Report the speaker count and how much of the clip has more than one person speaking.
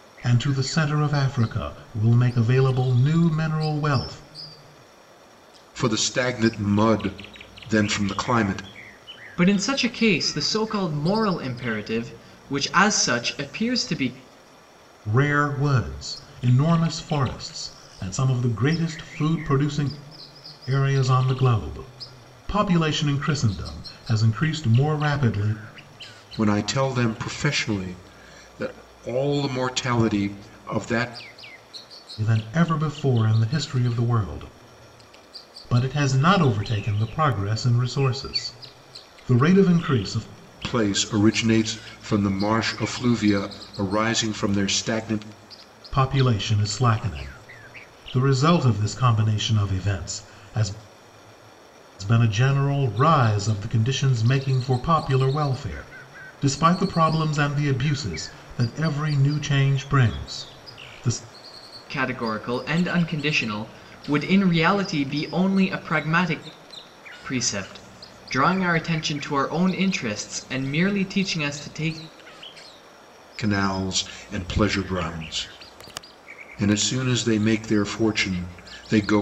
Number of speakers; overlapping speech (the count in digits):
3, no overlap